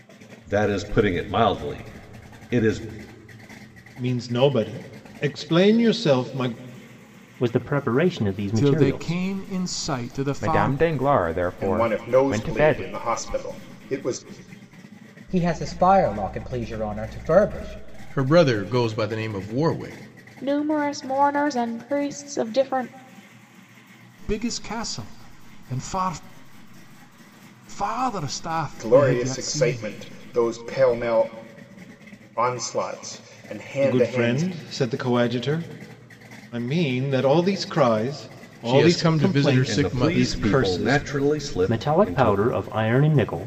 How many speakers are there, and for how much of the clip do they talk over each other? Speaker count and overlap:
9, about 17%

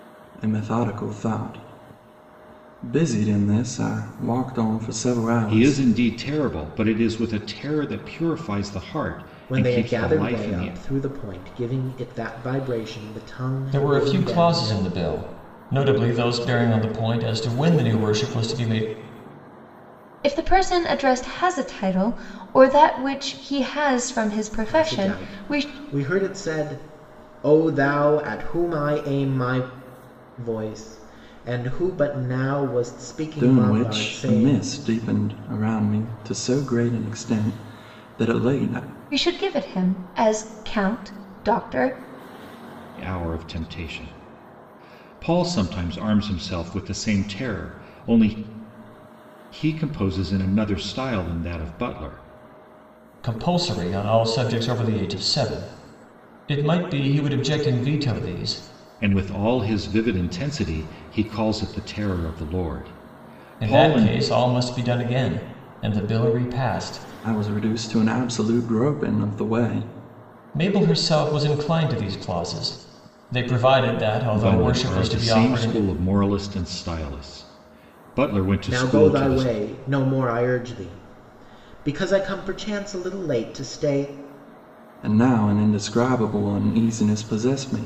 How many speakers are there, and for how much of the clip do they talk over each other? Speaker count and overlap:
5, about 9%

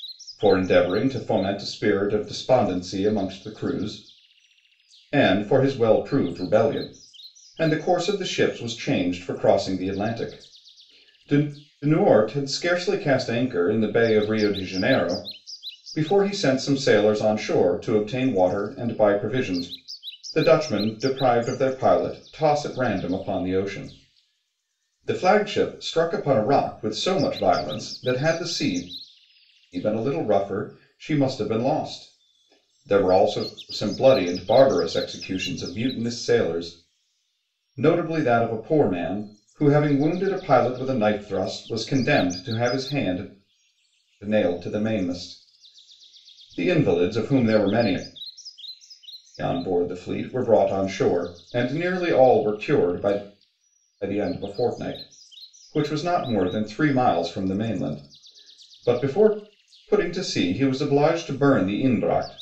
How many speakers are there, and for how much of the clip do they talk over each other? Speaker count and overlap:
1, no overlap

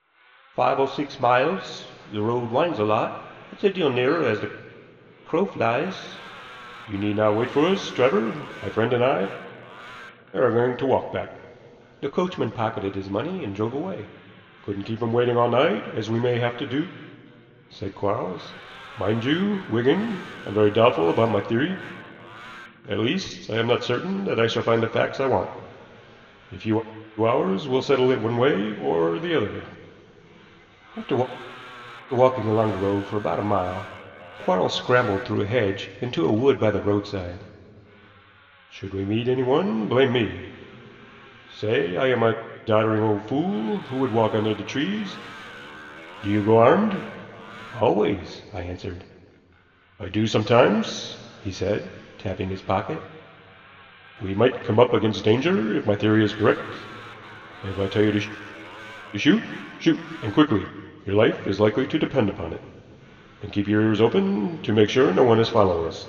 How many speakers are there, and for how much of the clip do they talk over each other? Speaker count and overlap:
1, no overlap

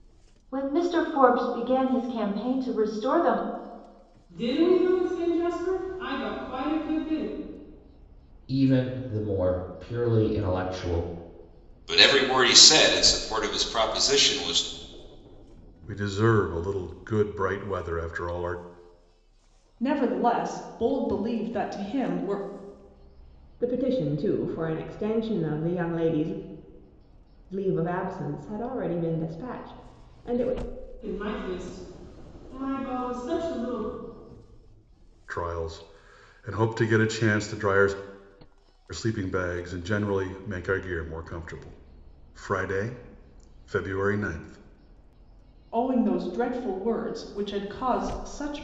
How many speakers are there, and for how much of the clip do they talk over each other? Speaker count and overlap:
7, no overlap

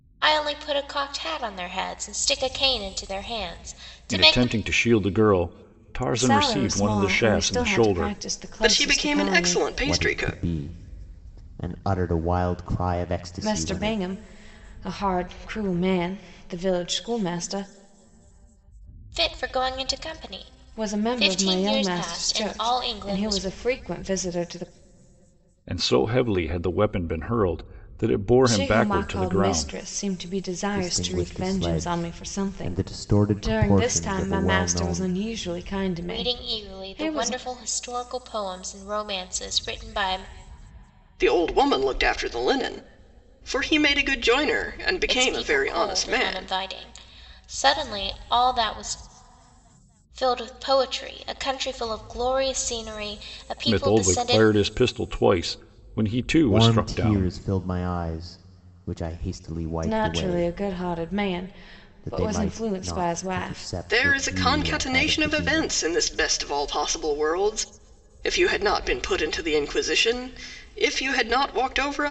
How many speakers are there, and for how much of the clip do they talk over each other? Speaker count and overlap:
5, about 31%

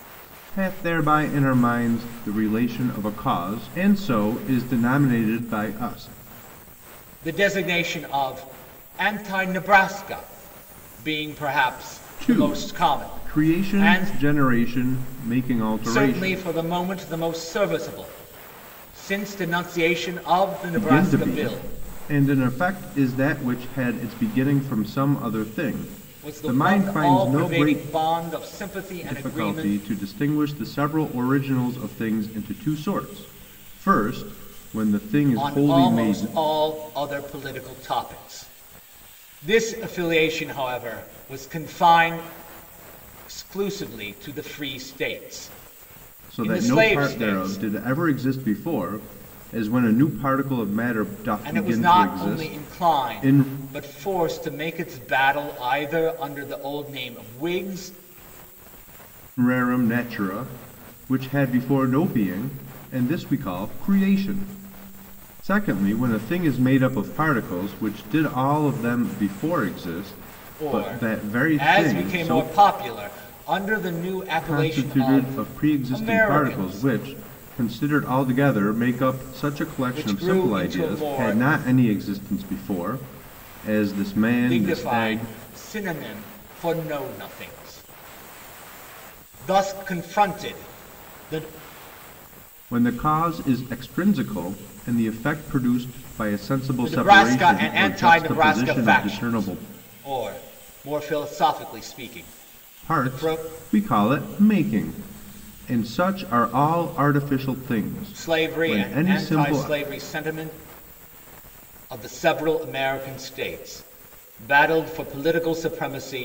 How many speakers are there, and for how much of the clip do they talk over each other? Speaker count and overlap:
2, about 19%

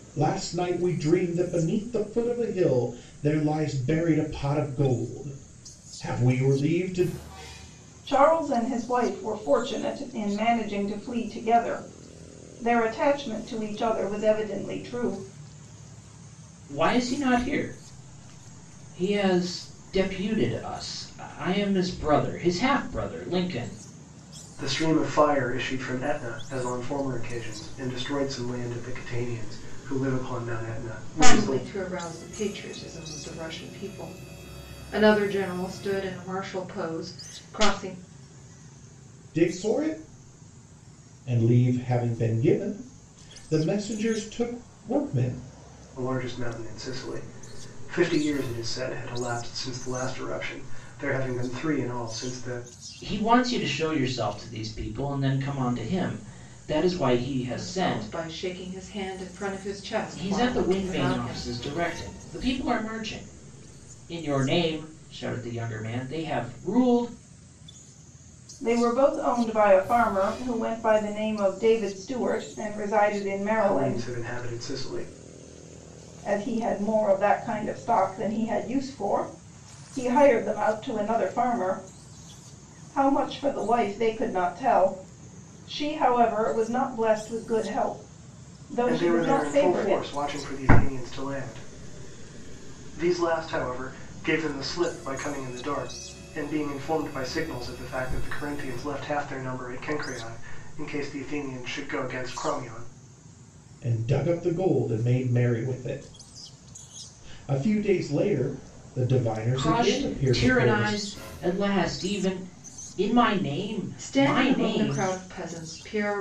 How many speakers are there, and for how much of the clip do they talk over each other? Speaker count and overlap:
5, about 6%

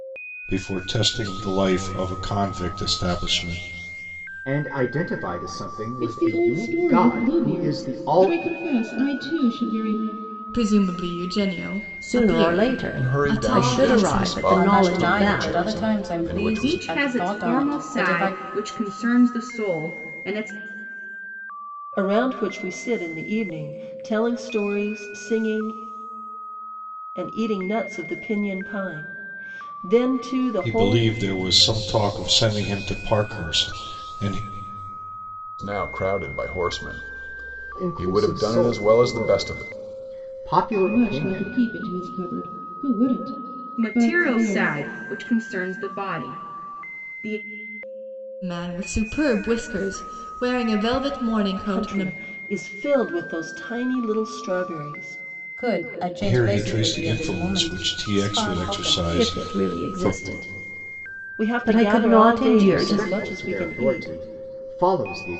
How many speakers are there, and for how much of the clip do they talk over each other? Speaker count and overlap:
9, about 31%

